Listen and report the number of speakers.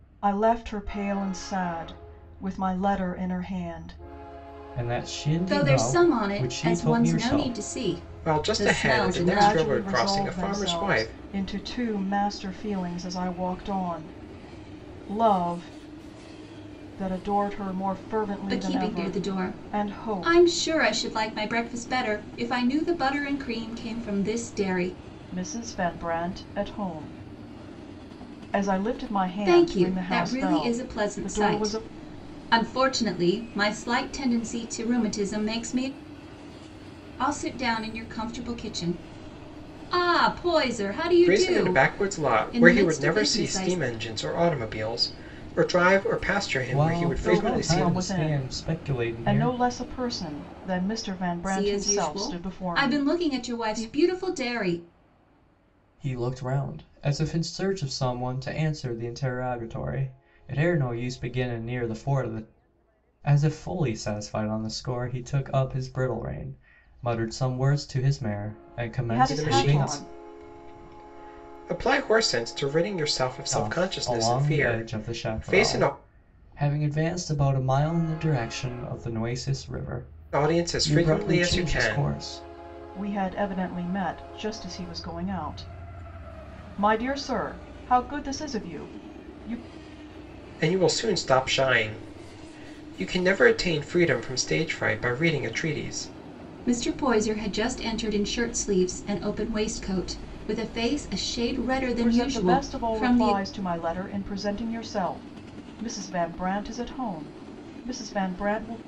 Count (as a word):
four